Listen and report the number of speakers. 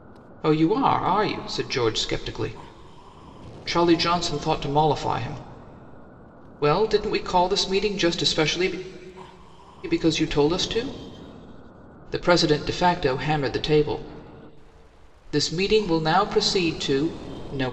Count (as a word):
one